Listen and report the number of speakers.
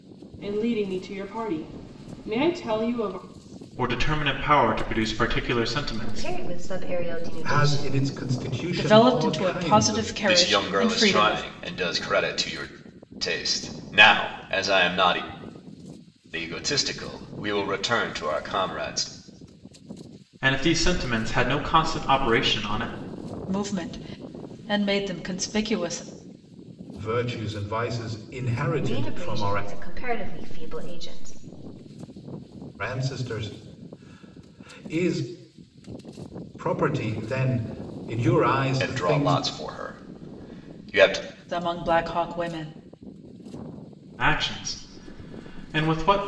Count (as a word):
six